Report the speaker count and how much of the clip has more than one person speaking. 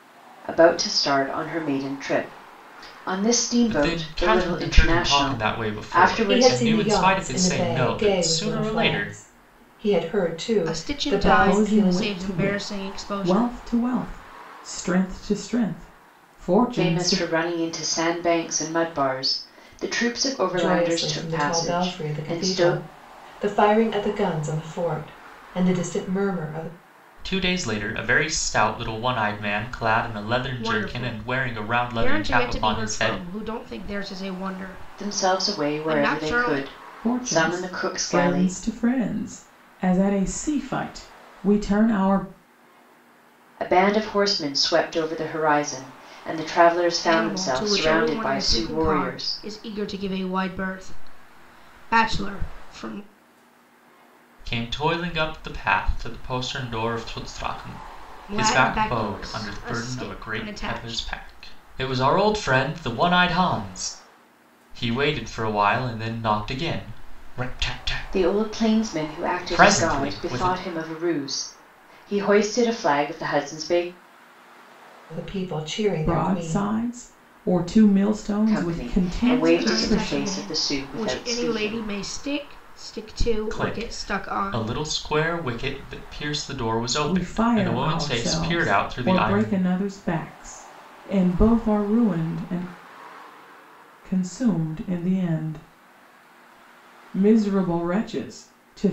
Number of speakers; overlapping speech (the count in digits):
5, about 33%